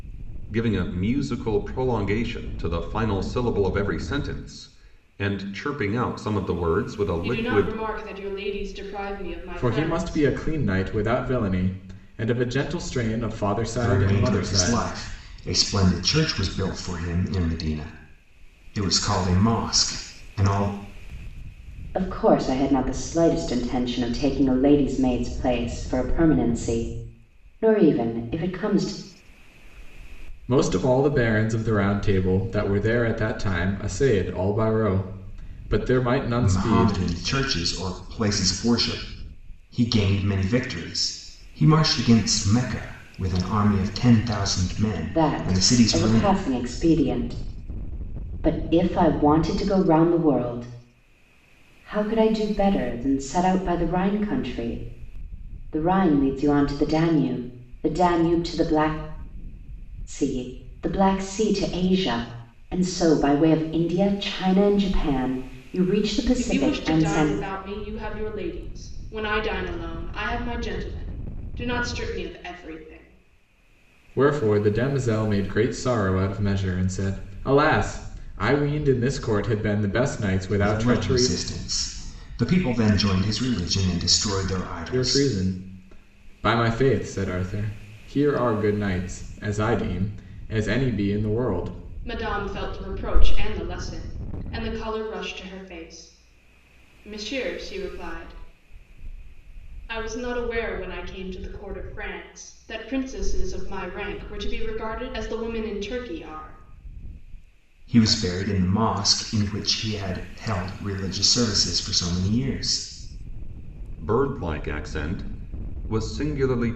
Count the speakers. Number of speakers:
5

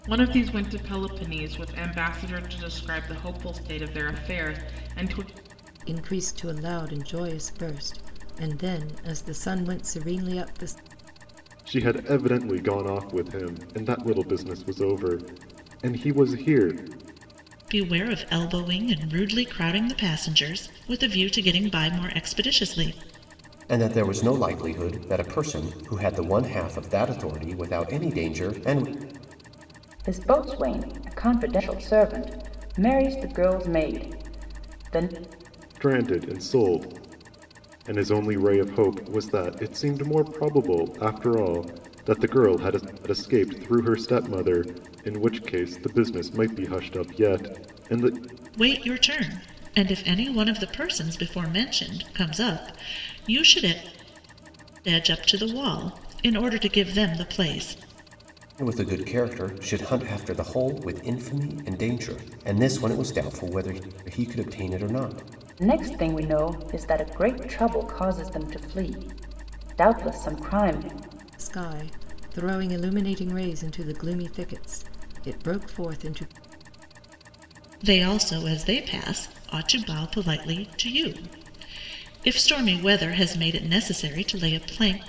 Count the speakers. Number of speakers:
6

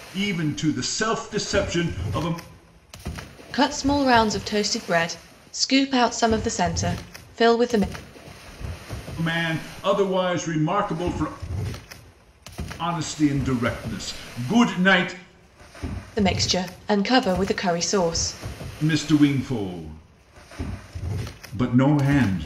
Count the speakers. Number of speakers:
2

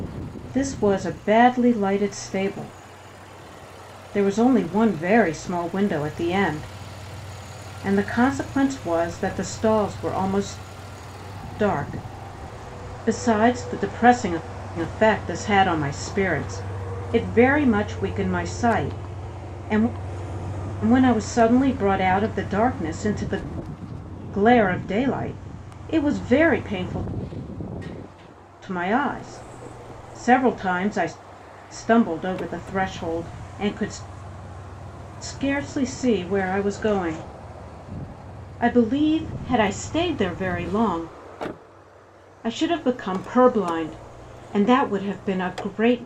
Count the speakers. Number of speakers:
1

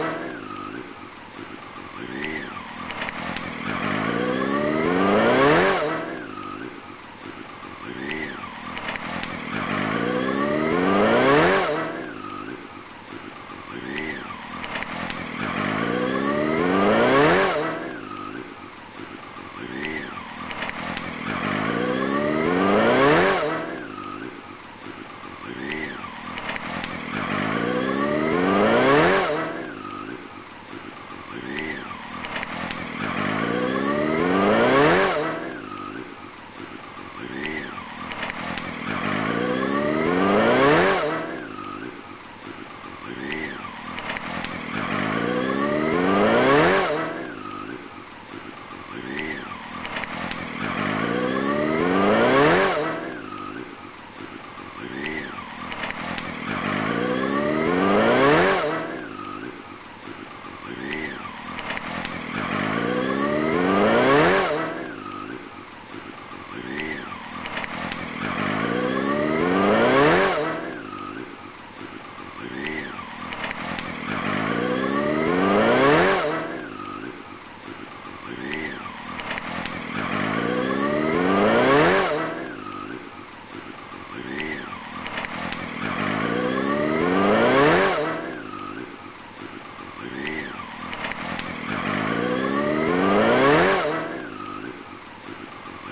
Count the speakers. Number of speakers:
0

